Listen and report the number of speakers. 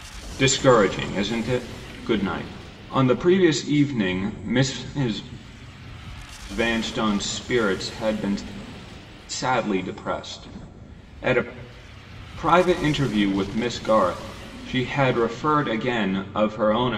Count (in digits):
1